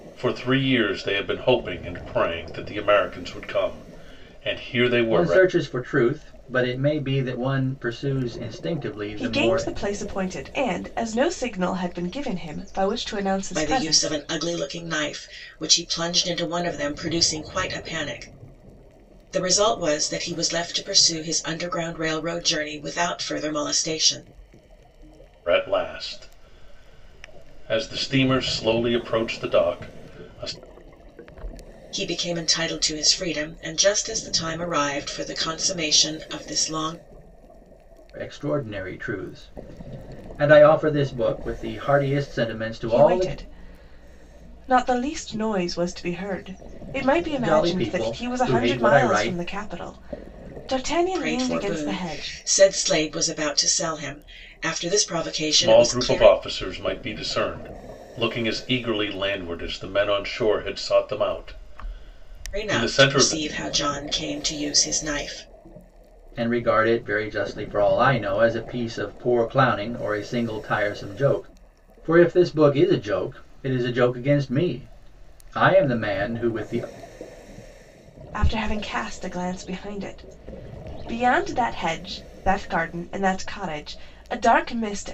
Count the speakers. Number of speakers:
4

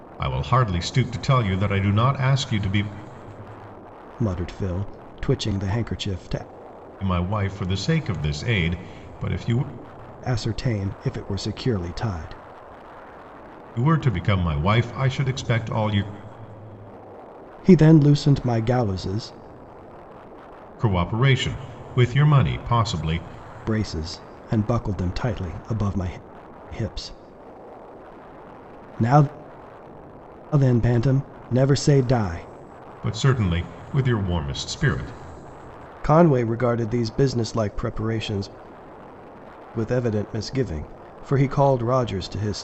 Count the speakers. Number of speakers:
2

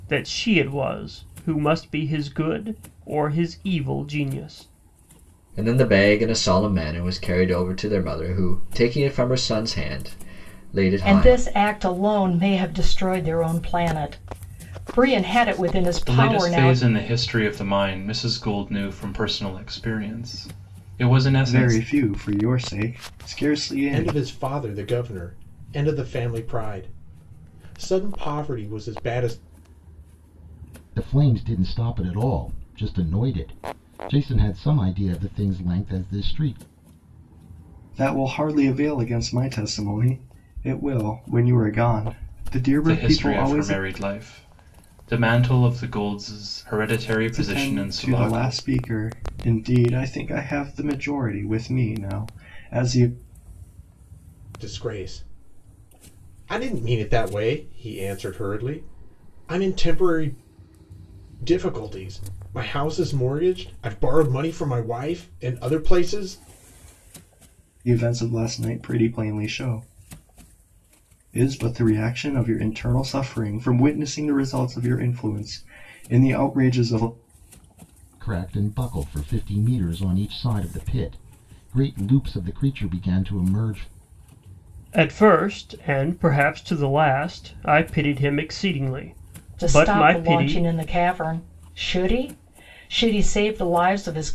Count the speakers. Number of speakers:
7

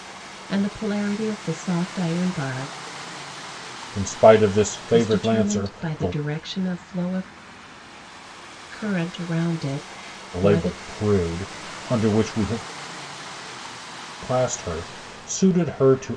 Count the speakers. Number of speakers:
2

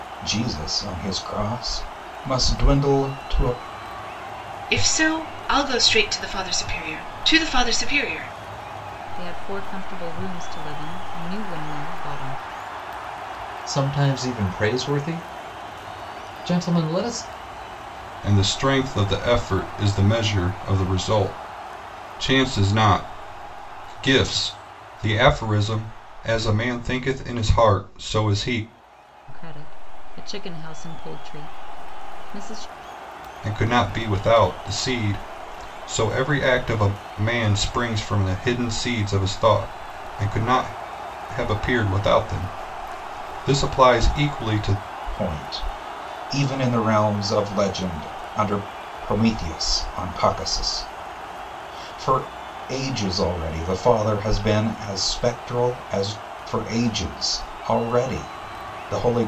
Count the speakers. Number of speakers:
5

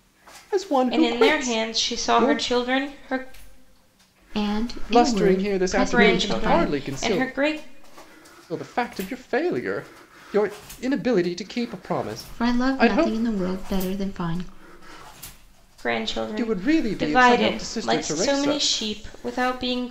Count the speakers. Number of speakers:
3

